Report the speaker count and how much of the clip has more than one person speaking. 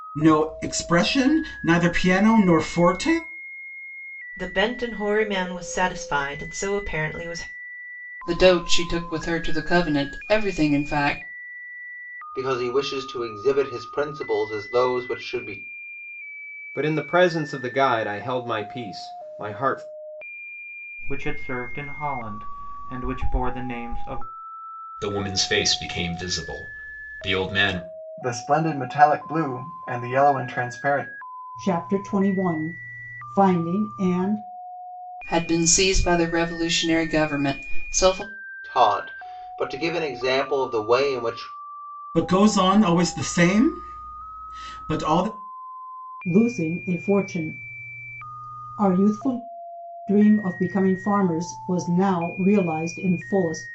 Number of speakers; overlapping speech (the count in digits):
9, no overlap